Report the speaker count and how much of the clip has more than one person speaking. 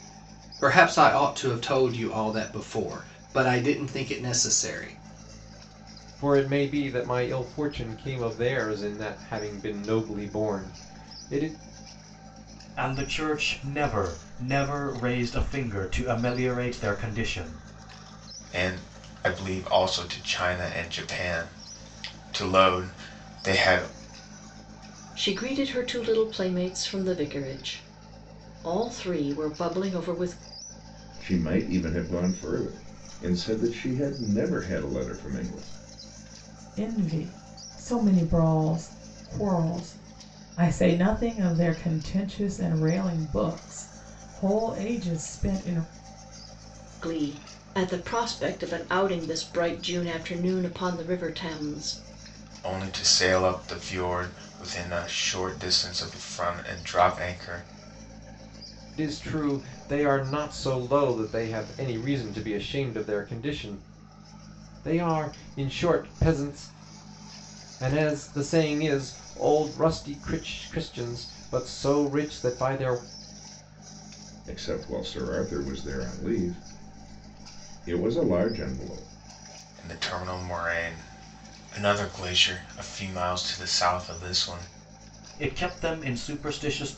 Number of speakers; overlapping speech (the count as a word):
seven, no overlap